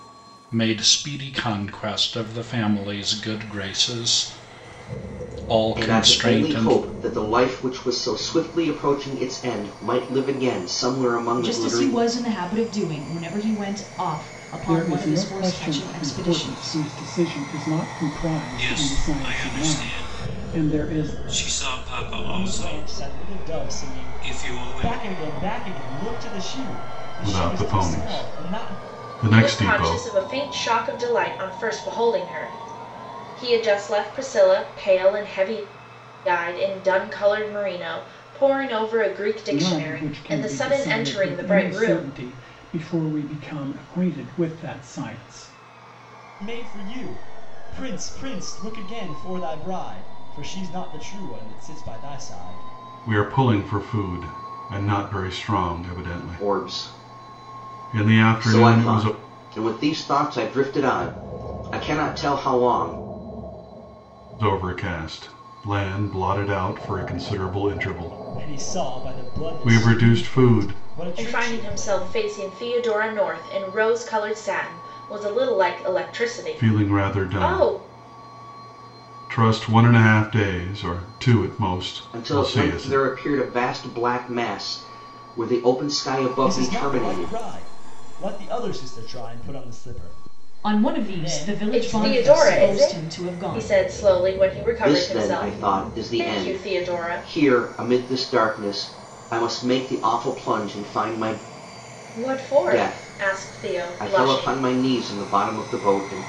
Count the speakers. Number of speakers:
8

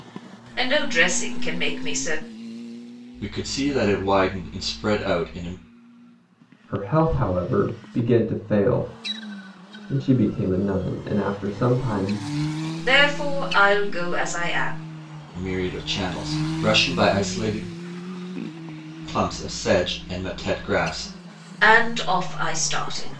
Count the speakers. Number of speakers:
3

